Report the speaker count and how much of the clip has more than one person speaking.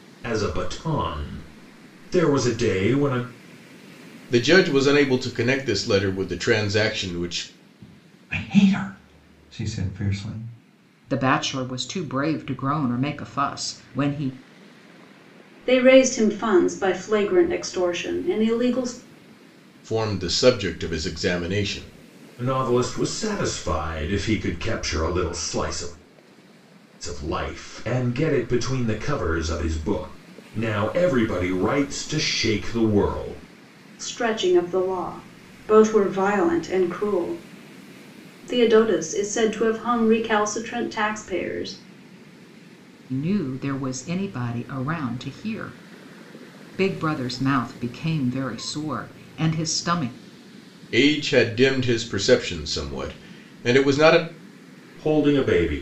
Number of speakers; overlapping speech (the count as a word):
five, no overlap